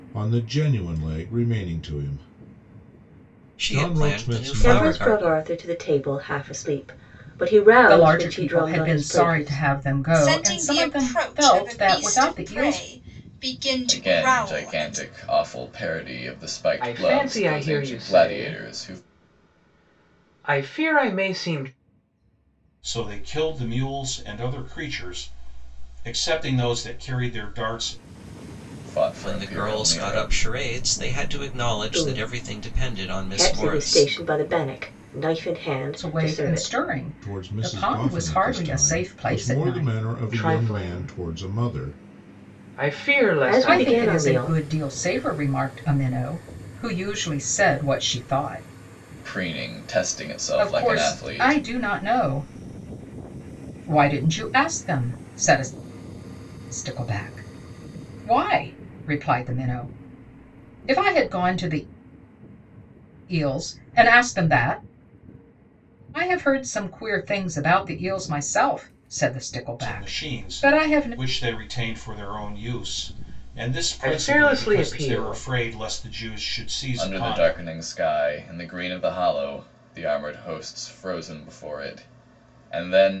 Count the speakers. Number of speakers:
8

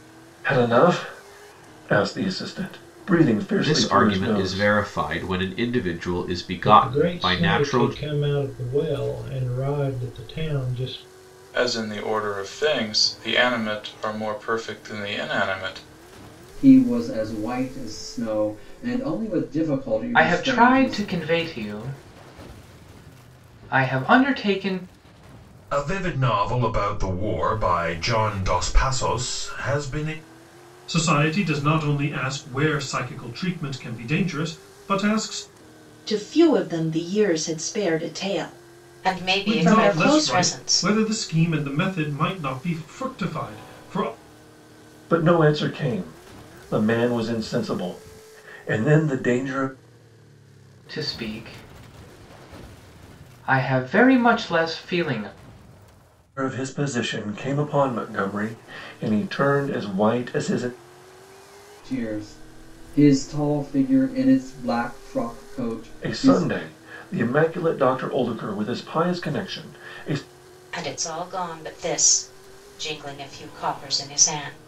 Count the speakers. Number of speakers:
10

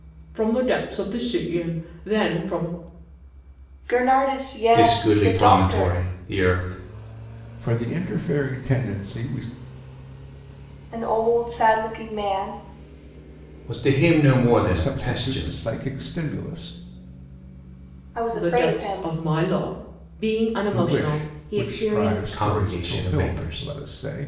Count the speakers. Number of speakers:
4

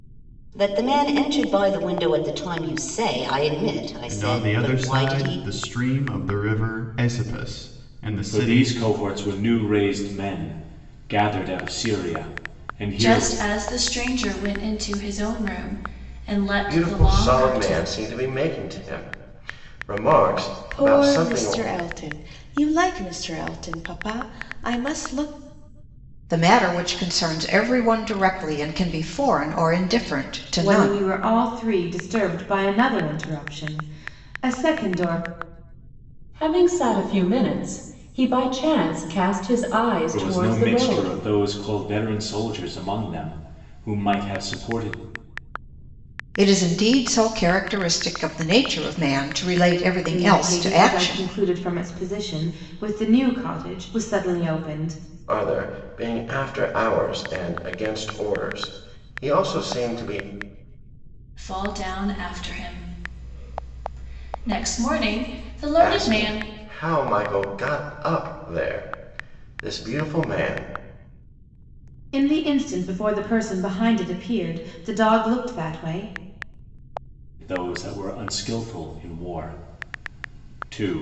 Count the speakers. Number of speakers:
9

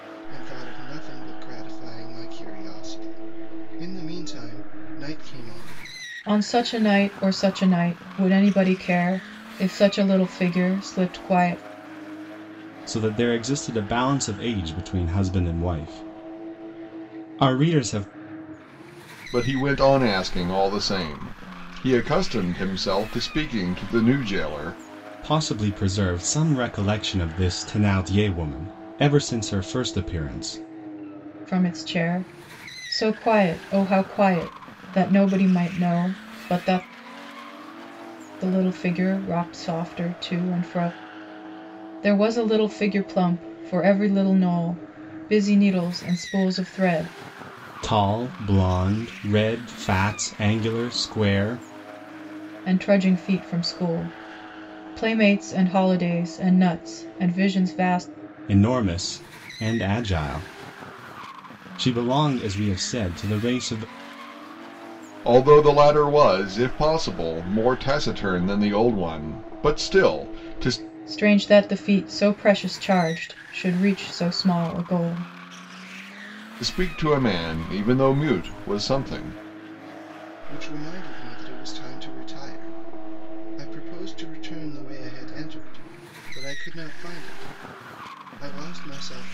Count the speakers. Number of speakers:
4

